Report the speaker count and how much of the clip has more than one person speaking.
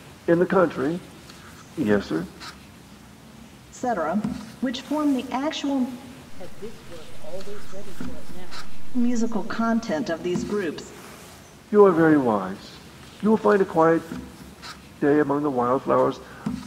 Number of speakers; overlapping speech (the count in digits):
3, no overlap